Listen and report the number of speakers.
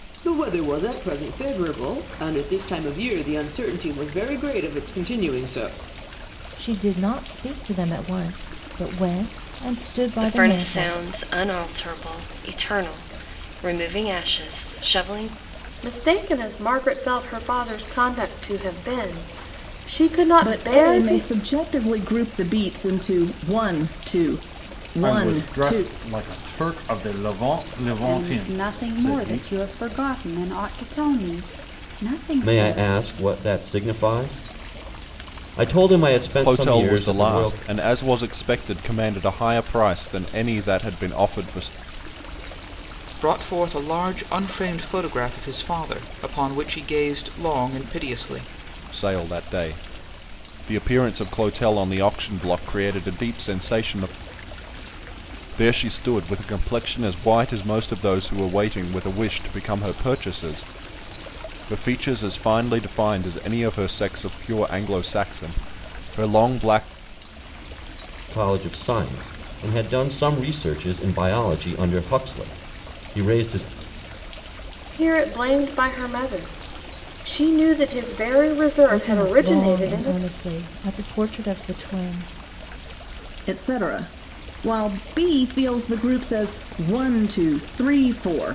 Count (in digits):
10